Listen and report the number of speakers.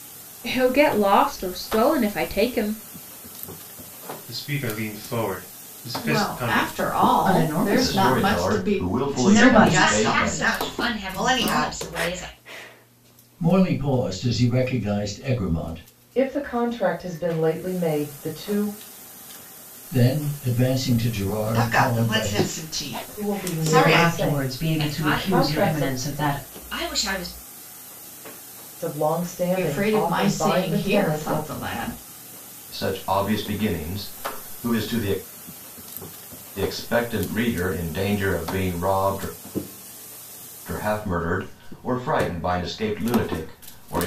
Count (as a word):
nine